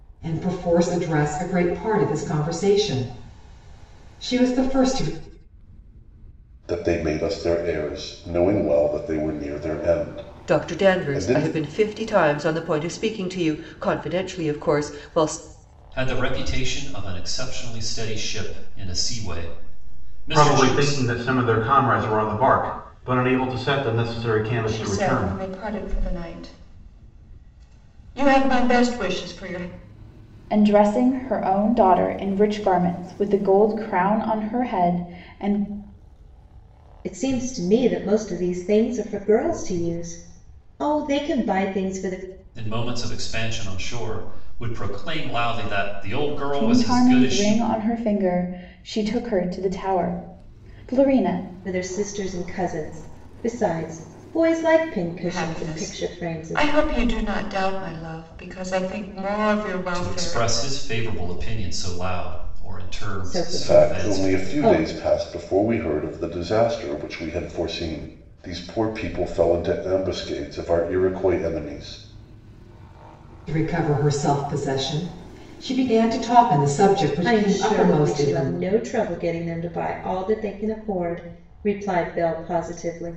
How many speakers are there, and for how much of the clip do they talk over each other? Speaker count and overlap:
eight, about 10%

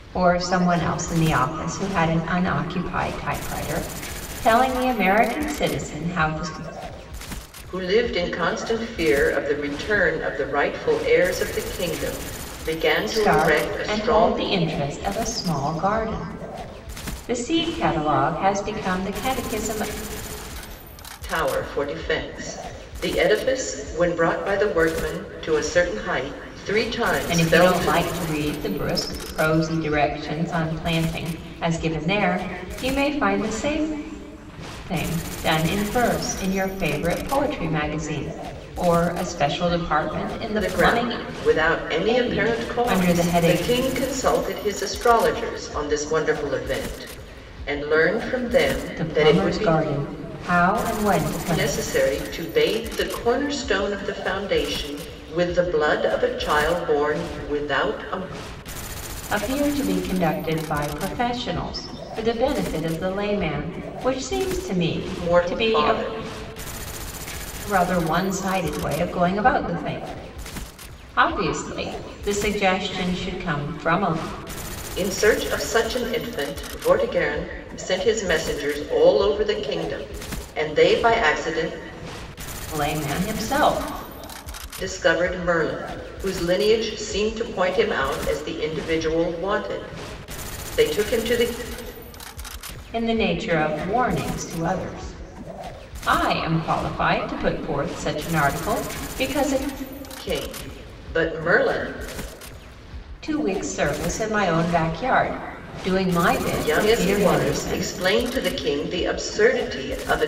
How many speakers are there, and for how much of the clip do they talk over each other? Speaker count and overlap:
two, about 7%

